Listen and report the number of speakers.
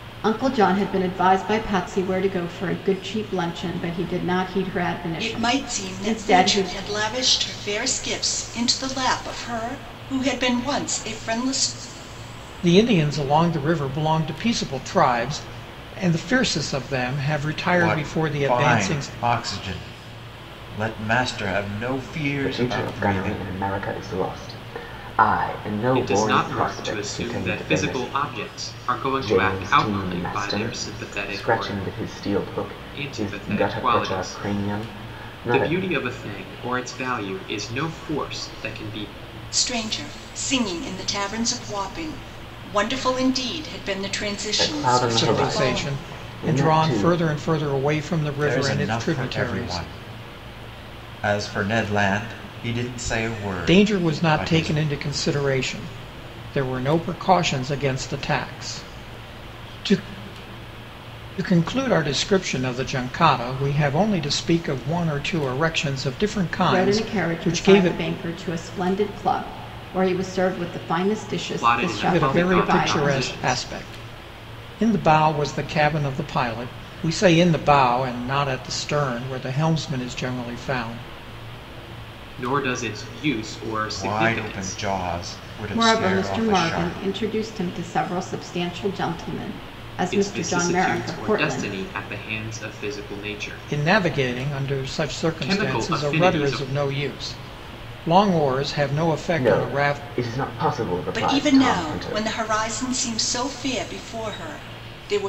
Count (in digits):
6